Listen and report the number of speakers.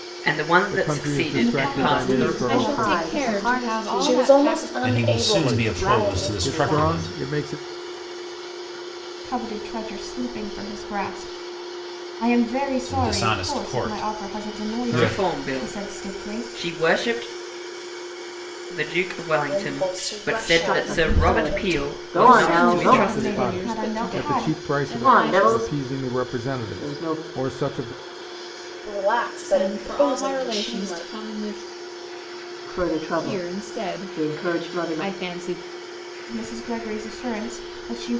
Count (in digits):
7